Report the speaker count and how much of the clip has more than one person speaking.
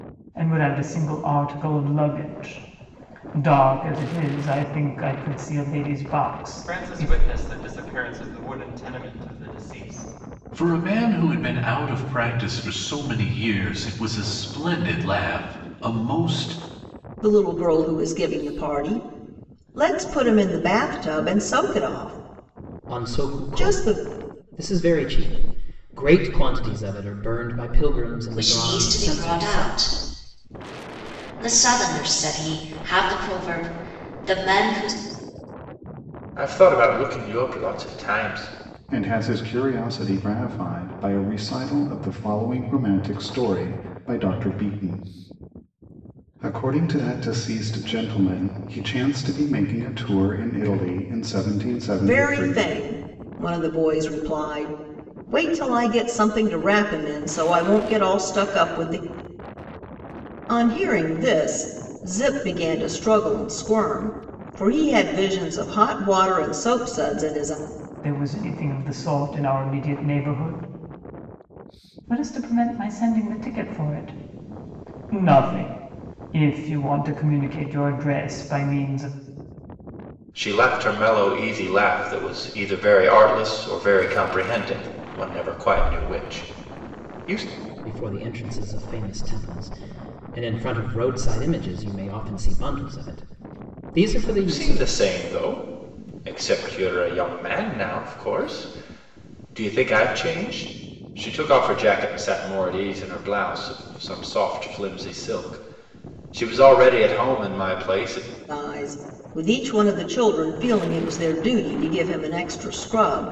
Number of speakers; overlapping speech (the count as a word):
eight, about 4%